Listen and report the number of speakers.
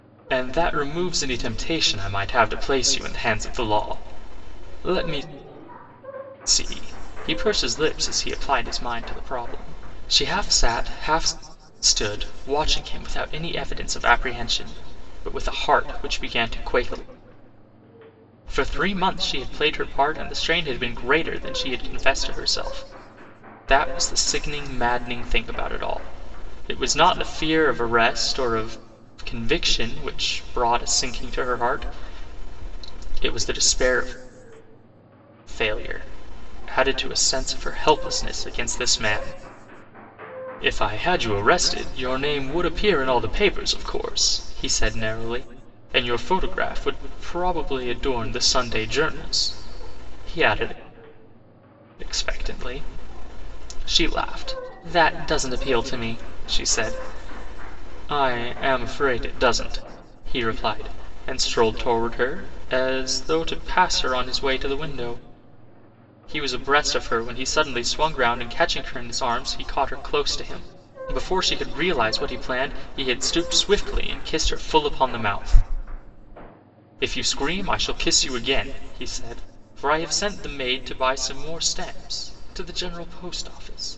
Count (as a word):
one